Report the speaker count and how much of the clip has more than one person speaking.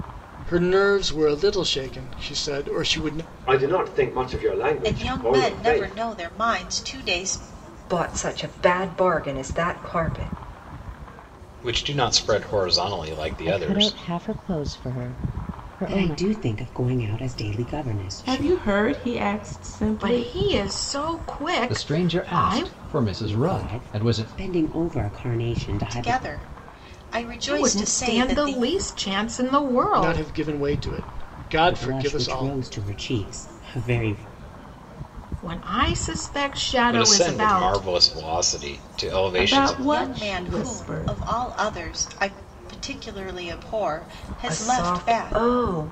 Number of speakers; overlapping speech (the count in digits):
10, about 25%